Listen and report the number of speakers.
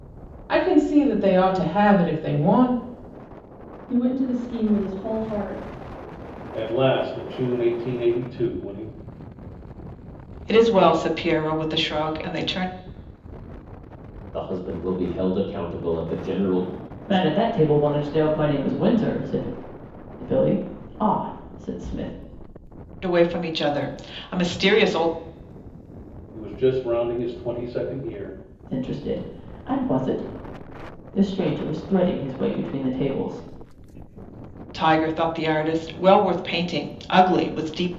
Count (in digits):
6